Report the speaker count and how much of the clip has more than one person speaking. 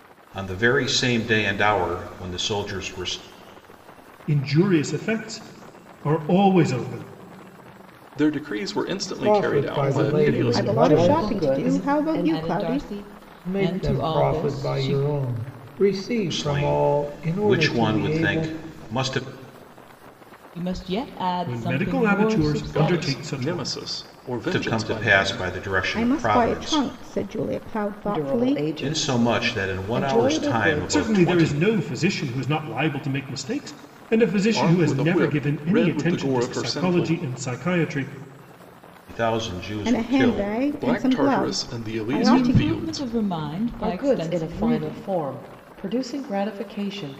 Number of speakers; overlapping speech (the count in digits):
7, about 47%